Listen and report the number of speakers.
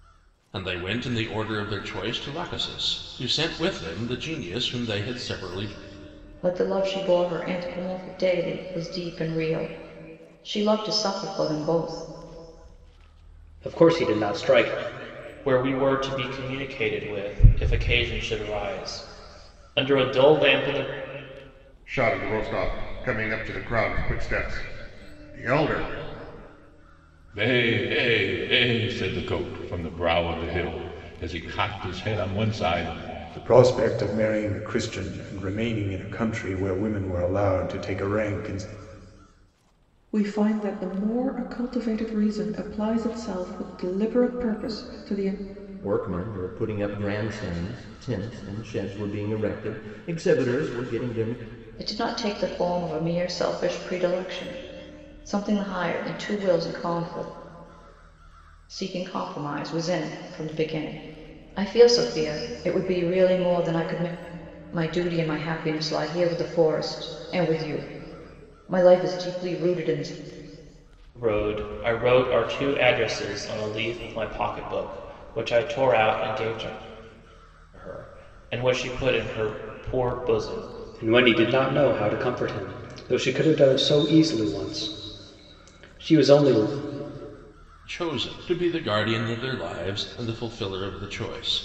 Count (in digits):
9